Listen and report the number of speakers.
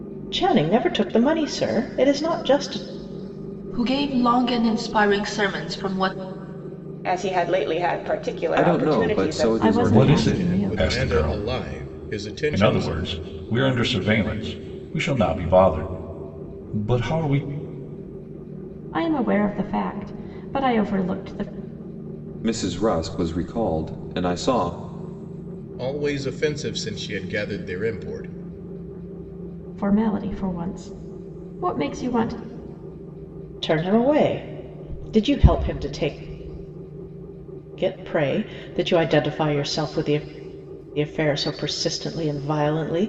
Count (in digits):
7